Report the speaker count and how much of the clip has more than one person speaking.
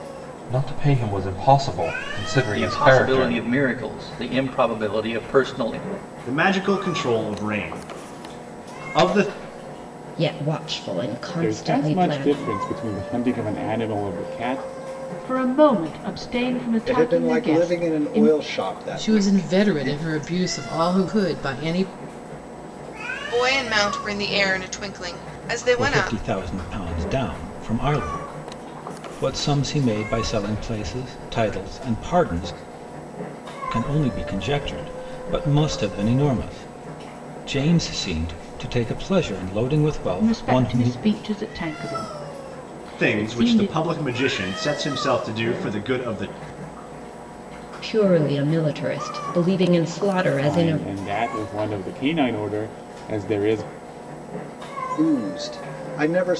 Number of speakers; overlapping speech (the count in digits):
10, about 13%